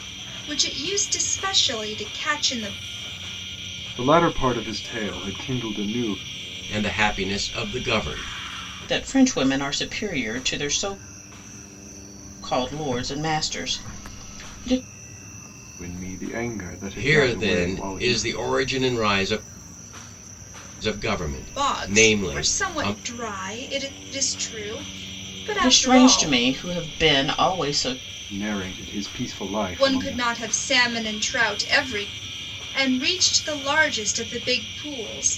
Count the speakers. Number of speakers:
four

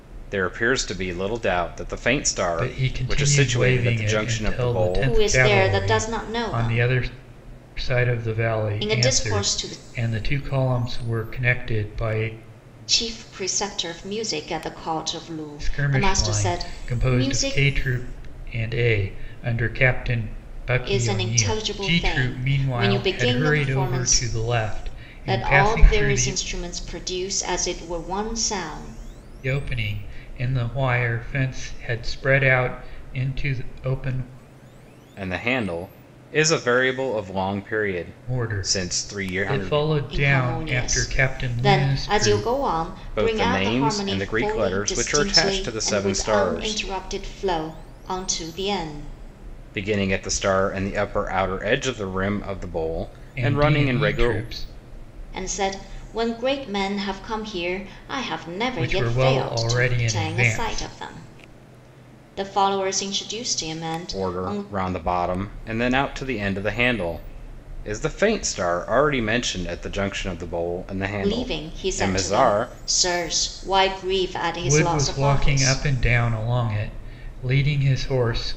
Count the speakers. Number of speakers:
three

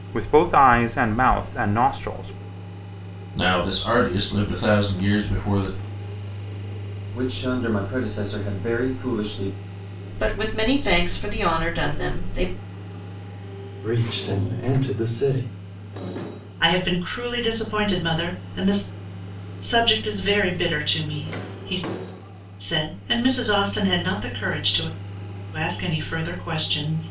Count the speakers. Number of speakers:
six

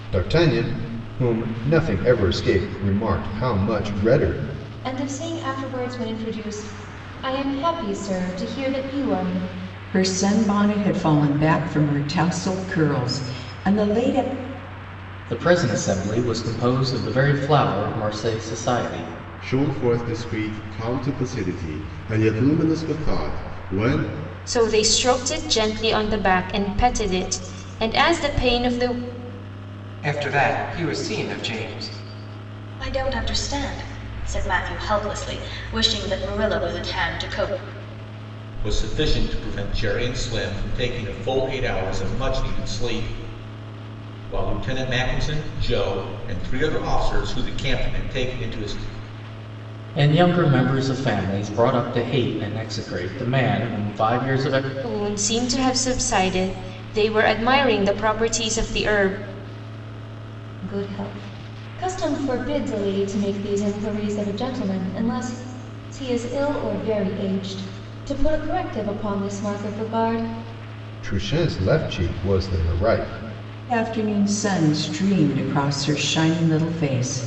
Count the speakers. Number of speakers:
nine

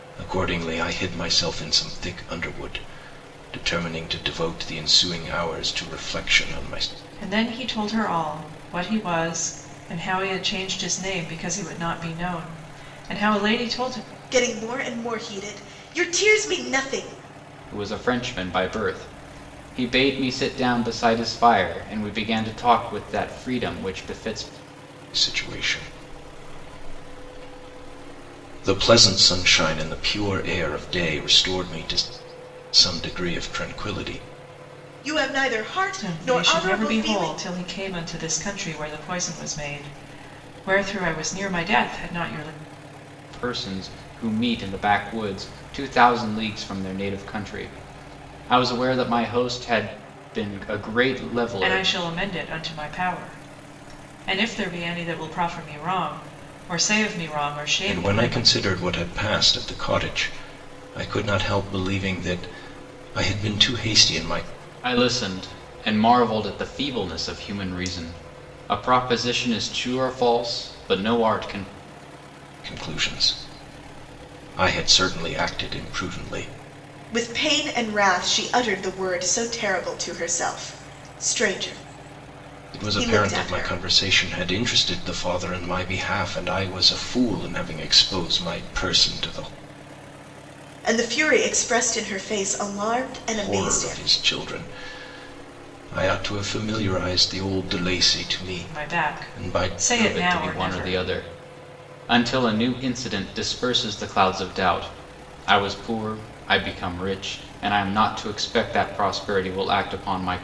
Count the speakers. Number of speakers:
four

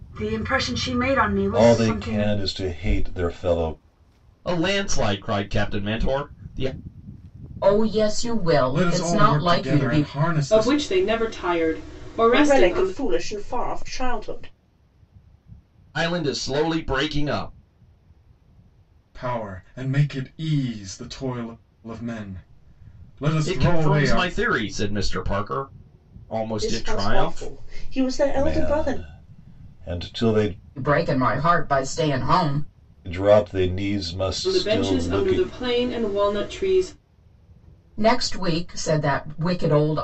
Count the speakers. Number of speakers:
seven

